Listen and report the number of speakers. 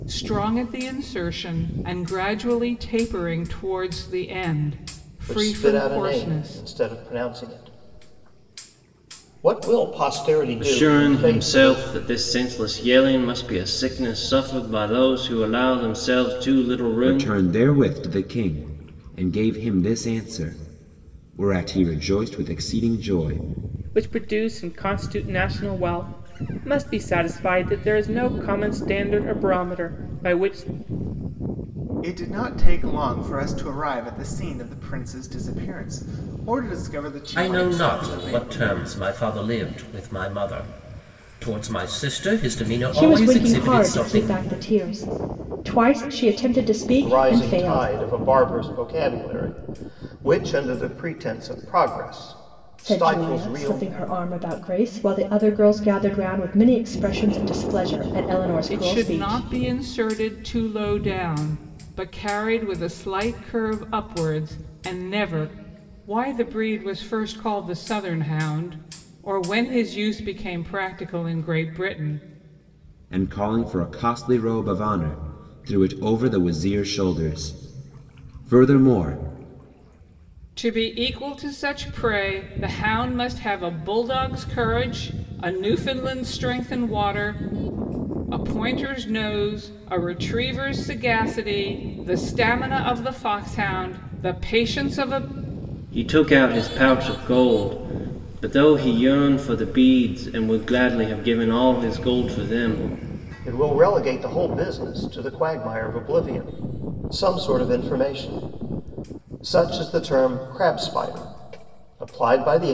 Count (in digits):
8